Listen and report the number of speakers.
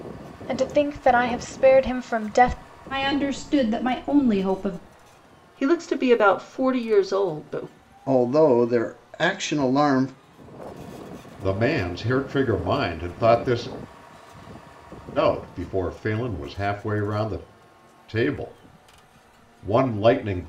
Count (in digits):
5